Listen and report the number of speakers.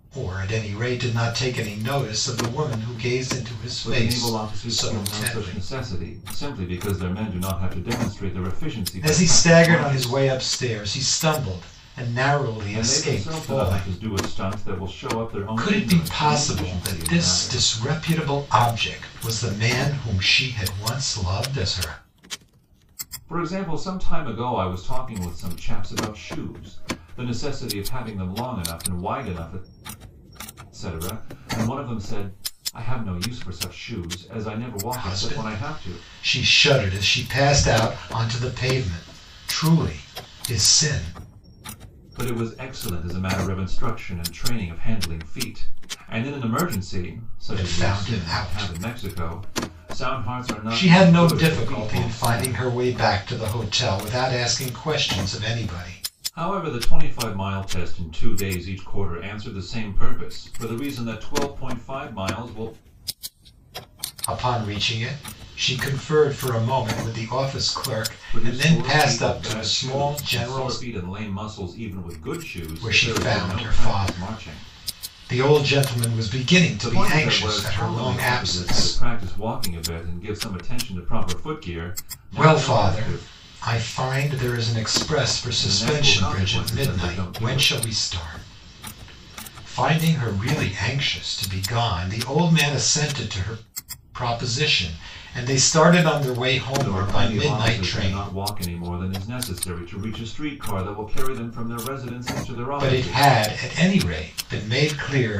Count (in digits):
2